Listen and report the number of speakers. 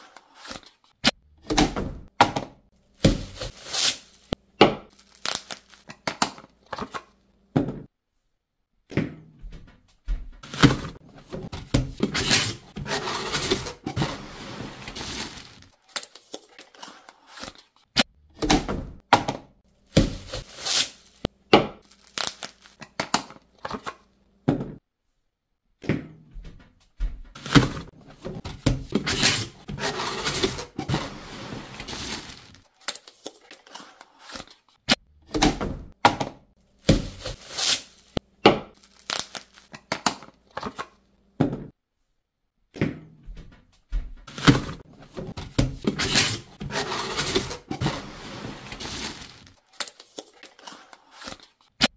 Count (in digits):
0